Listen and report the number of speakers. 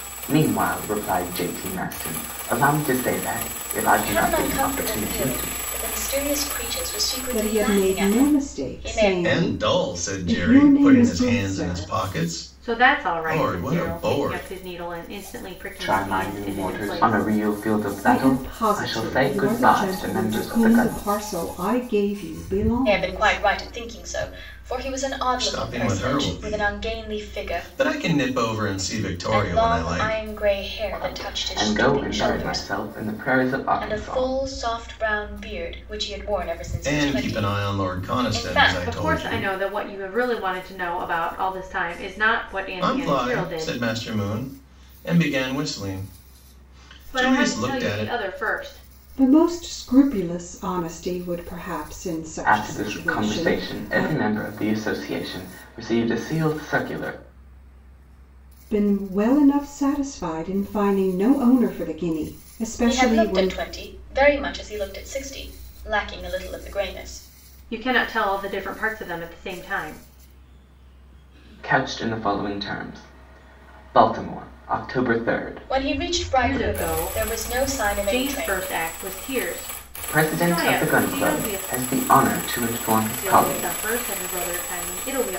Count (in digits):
5